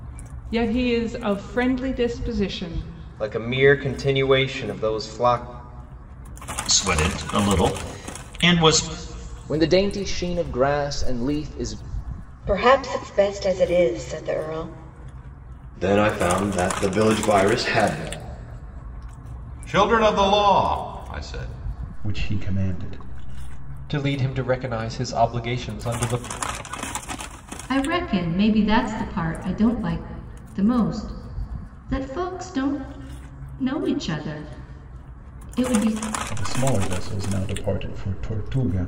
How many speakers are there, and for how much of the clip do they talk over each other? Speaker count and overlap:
10, no overlap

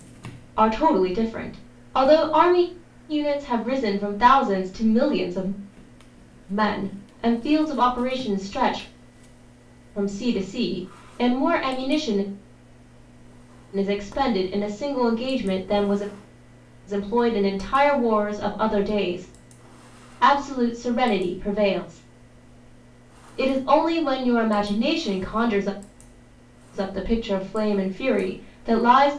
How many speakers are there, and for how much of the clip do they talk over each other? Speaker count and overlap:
1, no overlap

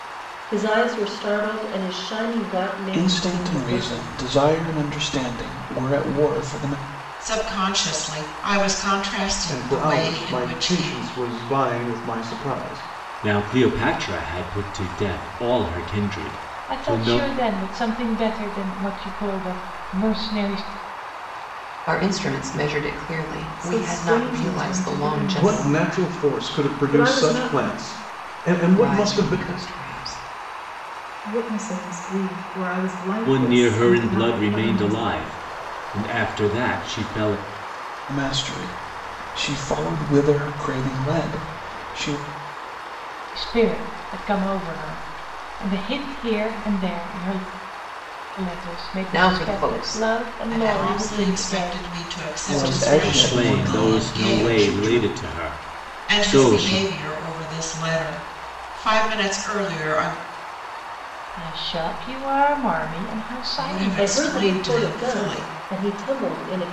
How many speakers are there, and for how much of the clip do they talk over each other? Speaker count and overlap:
8, about 28%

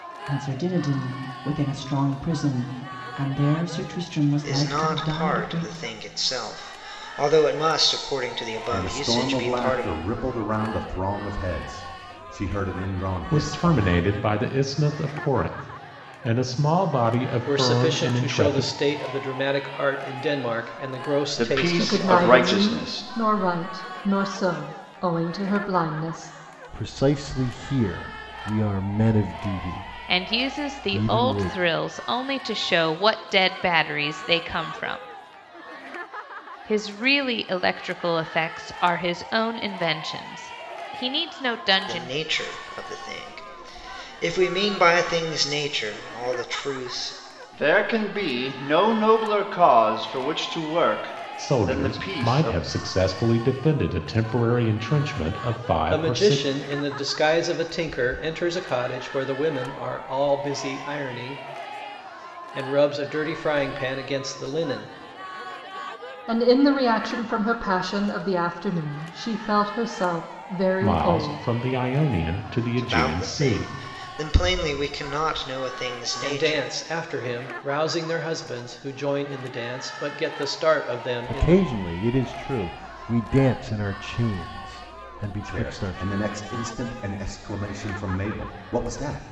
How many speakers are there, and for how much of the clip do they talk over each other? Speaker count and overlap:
9, about 15%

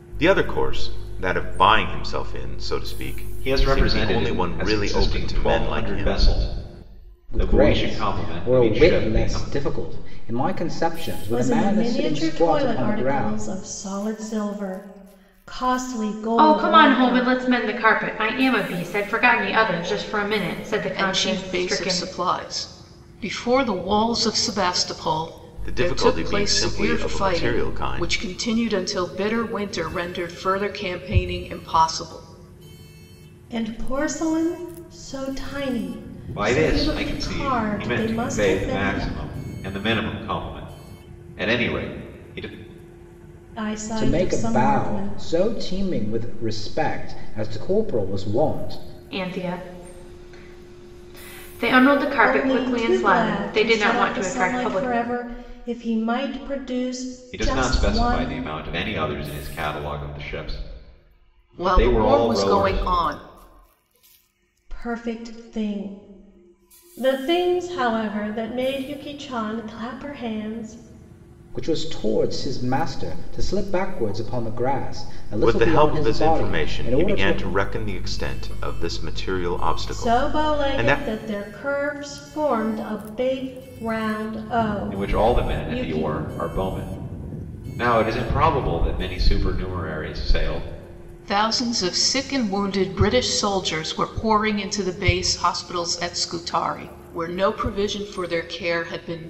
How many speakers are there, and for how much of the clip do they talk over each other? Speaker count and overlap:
6, about 26%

